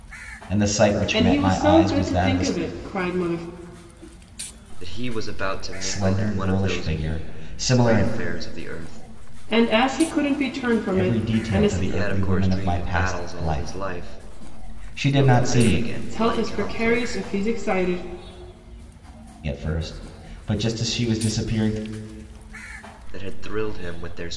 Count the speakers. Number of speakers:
3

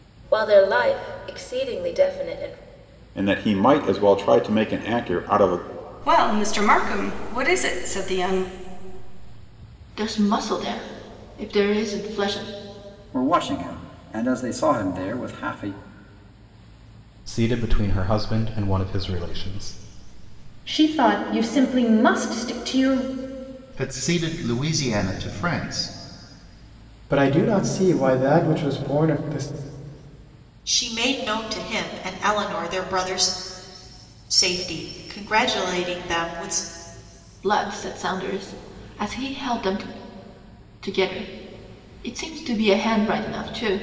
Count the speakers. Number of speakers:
10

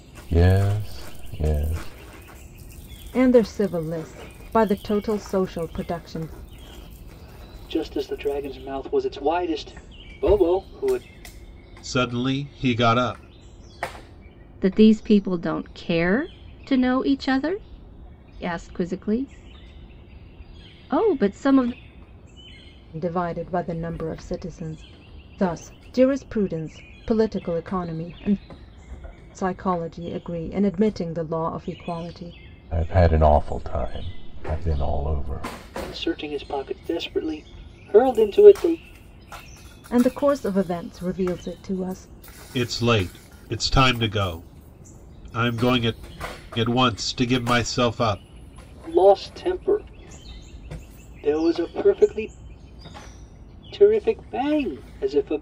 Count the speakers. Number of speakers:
5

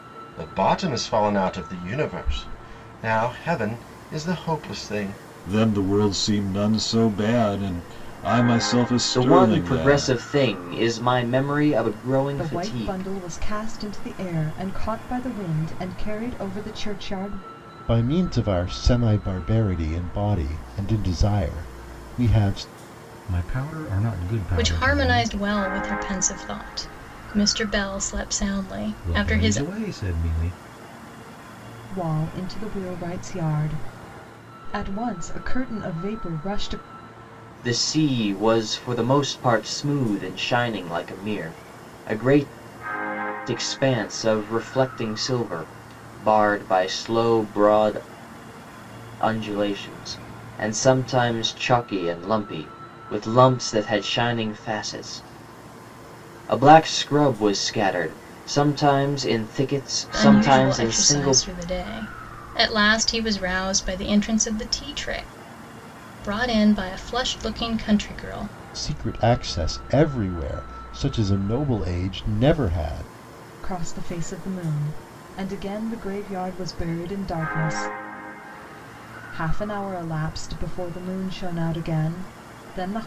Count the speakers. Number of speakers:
7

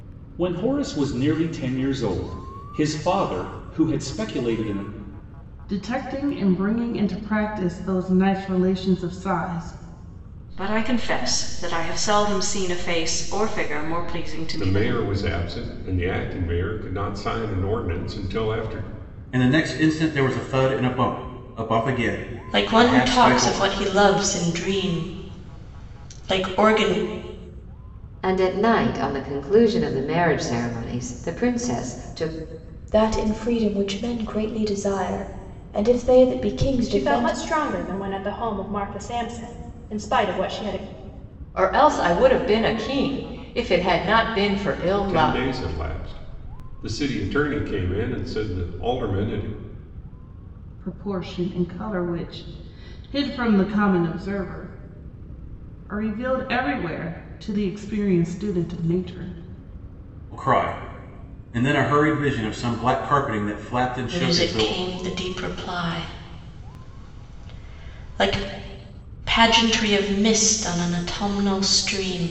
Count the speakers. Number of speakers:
10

